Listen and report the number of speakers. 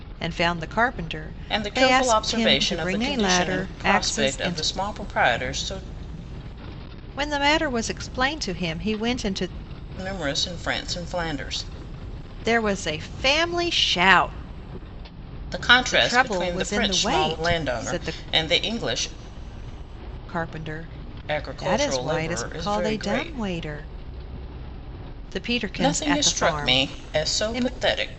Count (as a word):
two